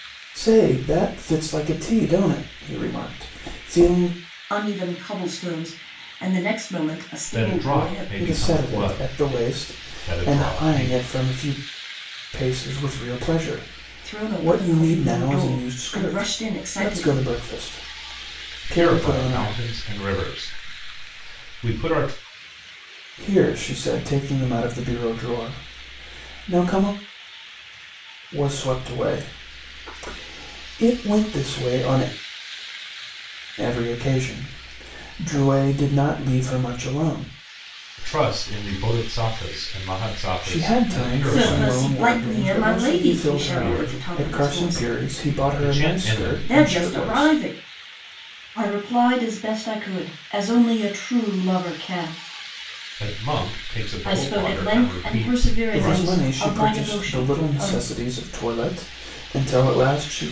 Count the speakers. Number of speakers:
3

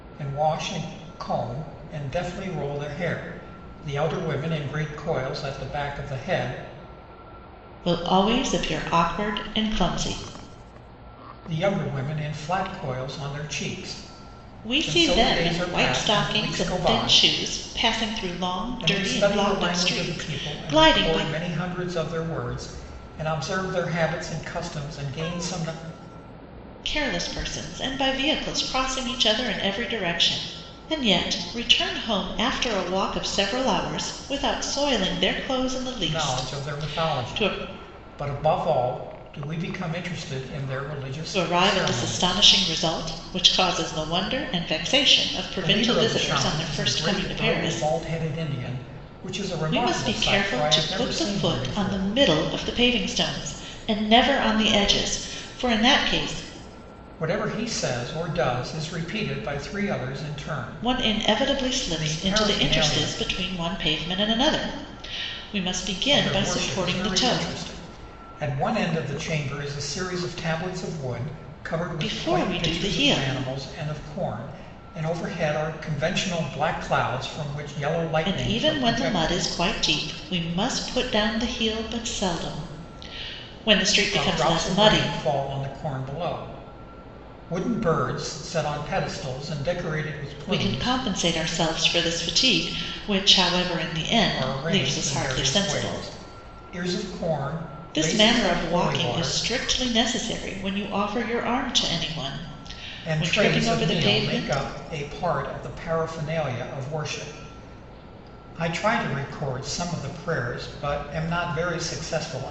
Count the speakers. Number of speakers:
2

